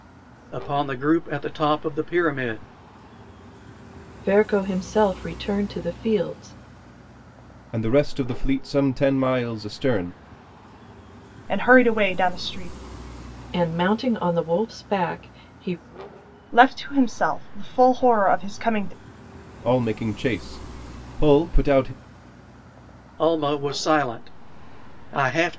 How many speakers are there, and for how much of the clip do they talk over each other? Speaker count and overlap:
four, no overlap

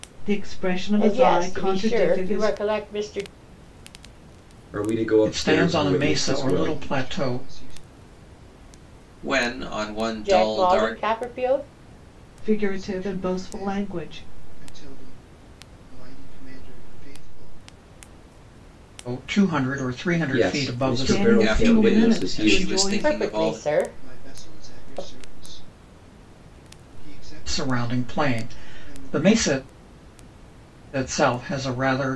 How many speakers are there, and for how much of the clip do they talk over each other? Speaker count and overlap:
six, about 39%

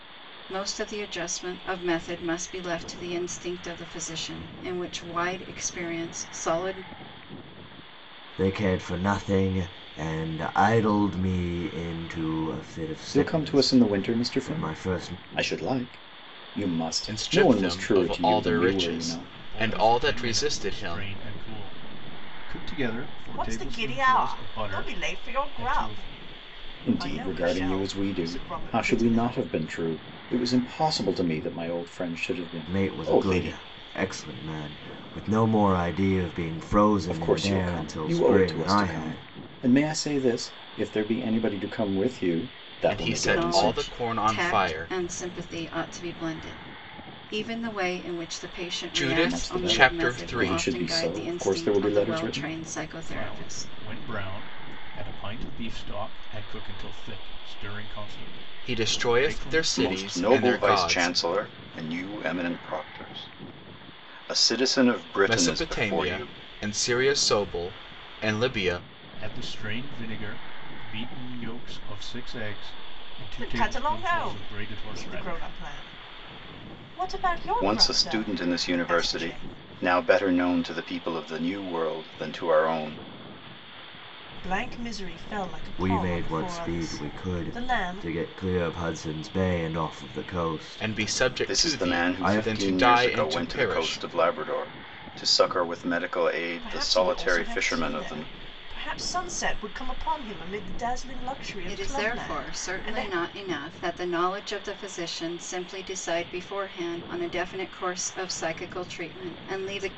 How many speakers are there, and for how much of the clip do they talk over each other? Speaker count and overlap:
six, about 34%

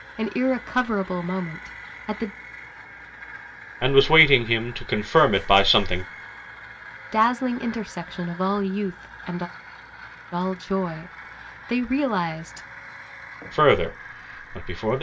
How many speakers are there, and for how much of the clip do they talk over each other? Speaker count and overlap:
two, no overlap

